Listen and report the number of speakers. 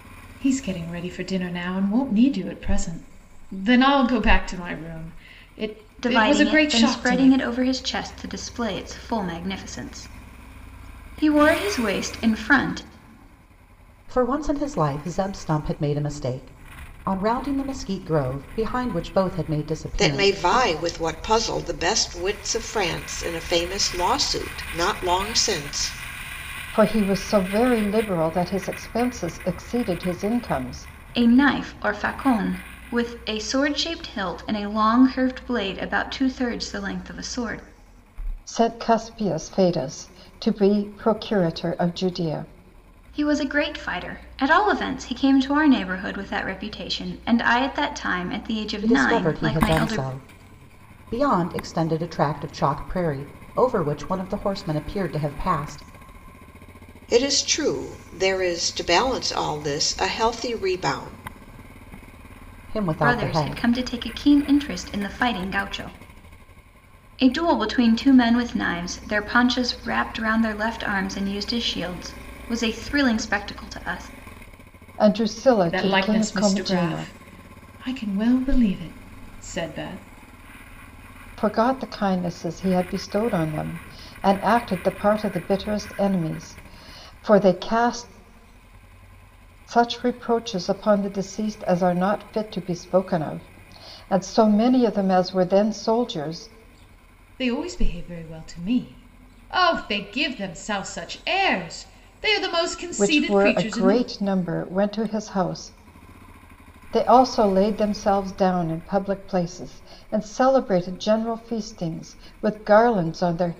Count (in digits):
5